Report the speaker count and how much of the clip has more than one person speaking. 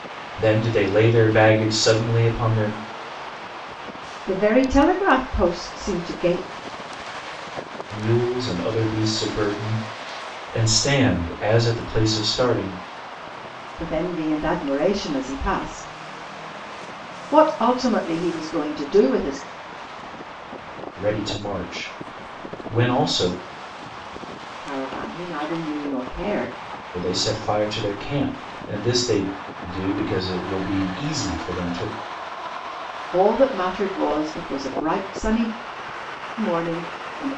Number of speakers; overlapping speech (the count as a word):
two, no overlap